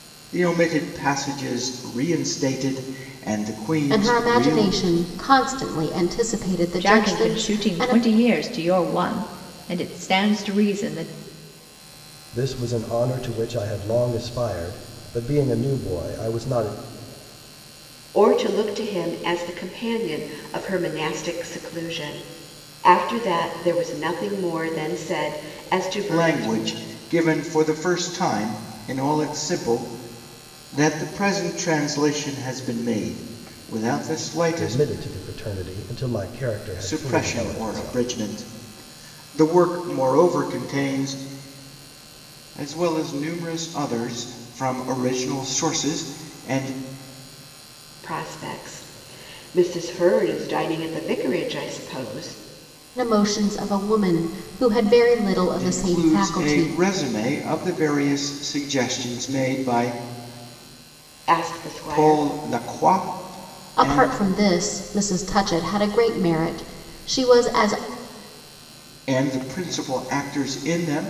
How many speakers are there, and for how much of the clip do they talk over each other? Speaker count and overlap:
5, about 9%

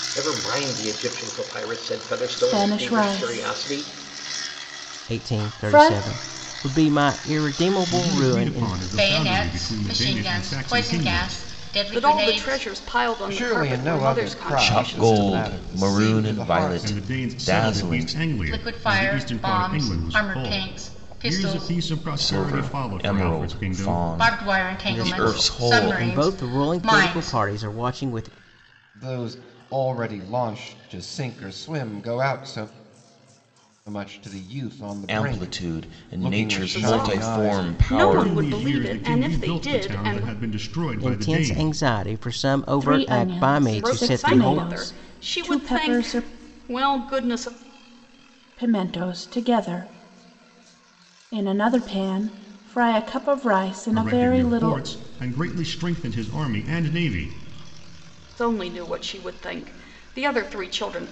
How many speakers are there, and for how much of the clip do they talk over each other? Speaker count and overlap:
8, about 50%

